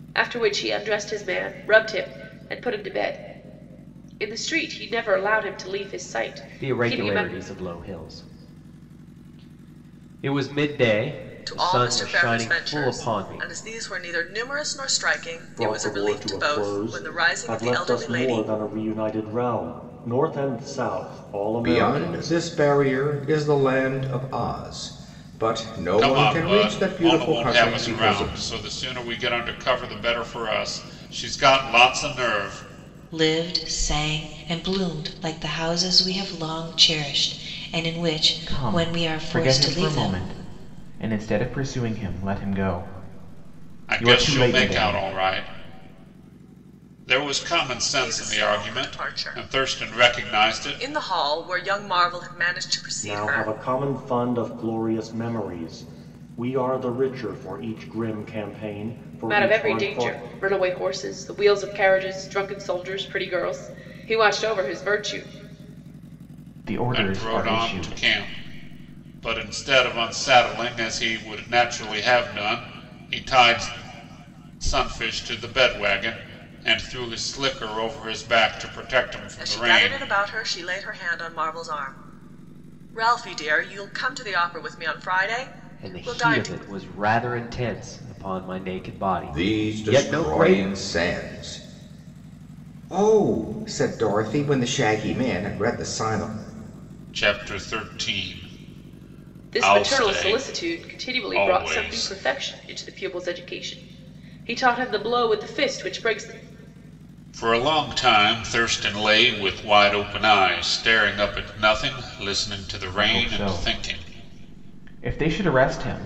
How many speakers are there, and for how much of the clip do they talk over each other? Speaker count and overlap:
eight, about 21%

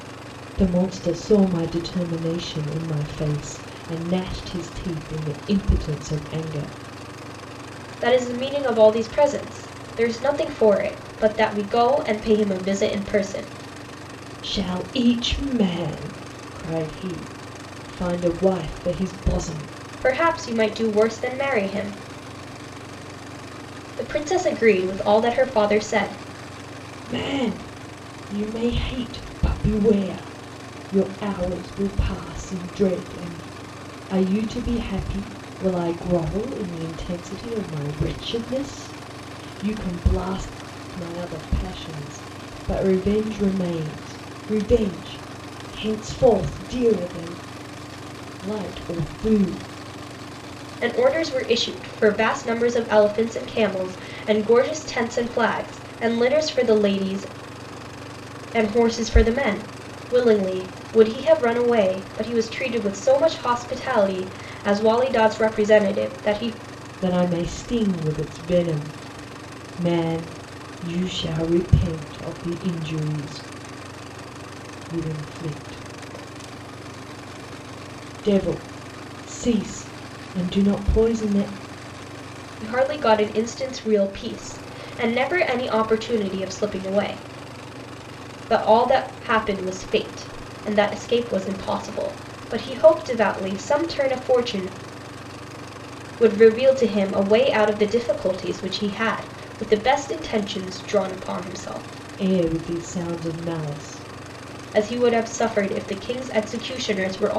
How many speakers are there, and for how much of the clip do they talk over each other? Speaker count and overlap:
two, no overlap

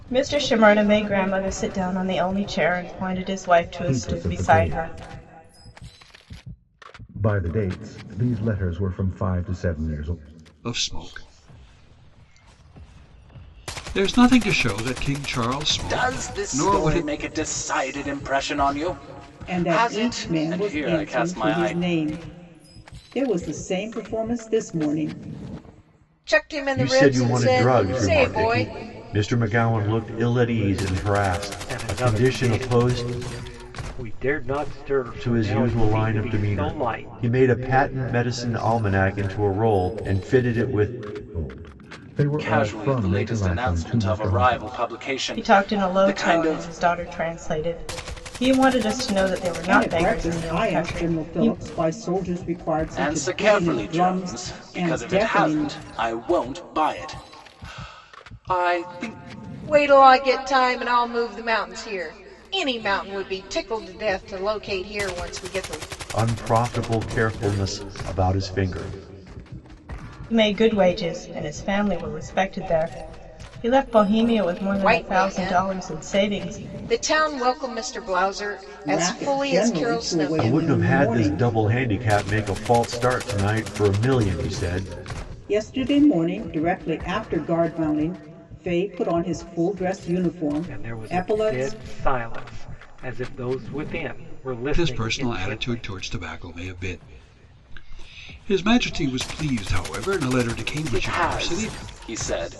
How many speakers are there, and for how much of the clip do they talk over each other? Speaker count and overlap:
eight, about 26%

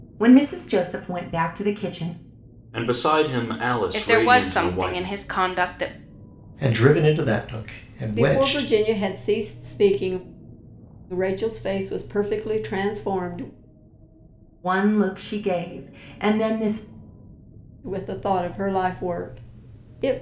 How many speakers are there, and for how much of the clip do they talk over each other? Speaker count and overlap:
five, about 9%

